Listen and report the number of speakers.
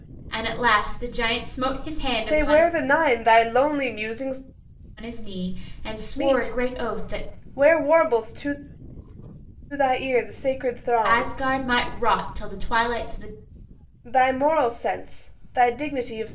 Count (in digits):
2